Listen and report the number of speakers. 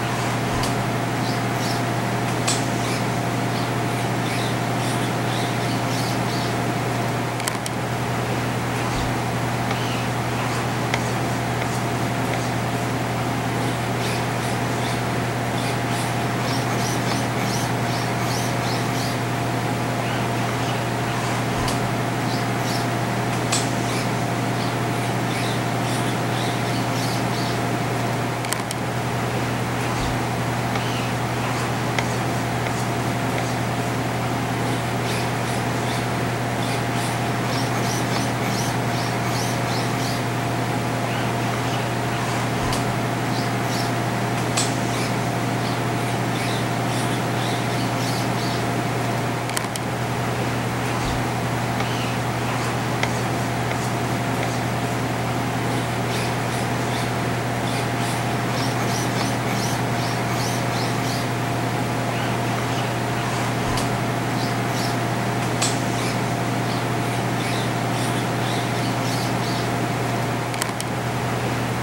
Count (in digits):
0